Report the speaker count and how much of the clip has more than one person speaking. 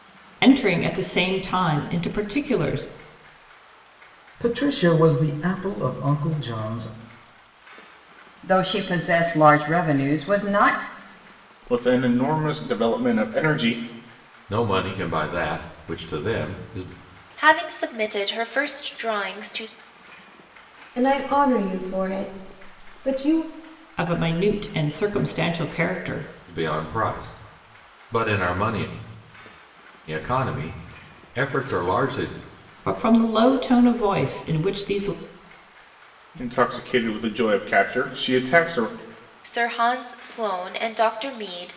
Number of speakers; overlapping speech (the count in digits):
7, no overlap